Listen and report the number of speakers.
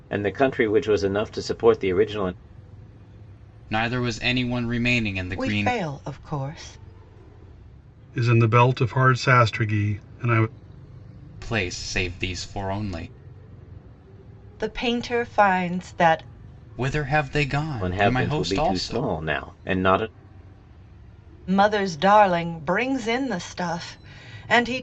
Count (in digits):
4